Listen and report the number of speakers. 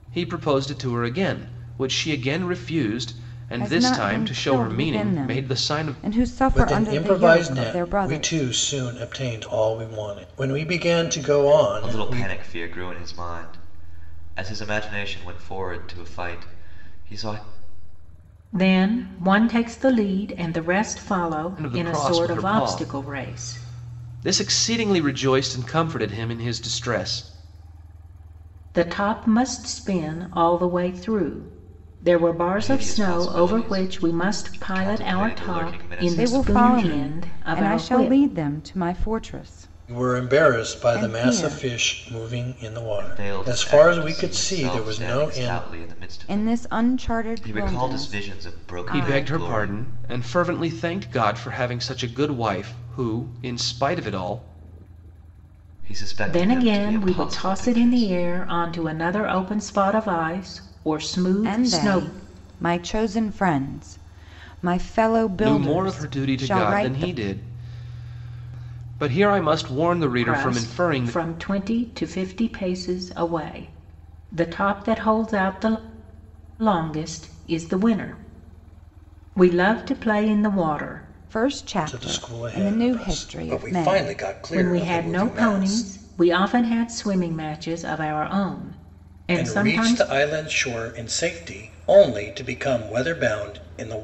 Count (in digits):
5